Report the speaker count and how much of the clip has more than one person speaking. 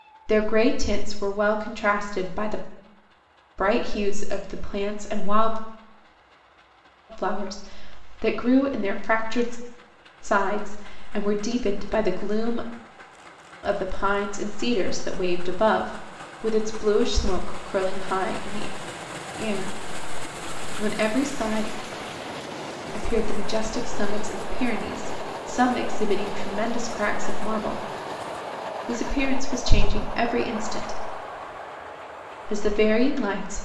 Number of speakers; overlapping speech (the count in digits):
1, no overlap